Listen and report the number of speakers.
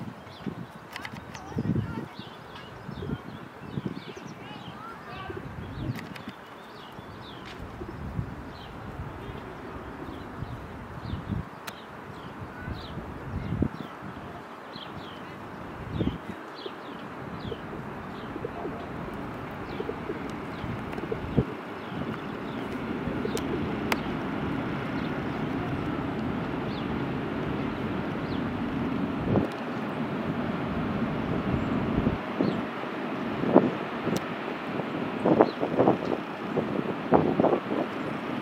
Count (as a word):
zero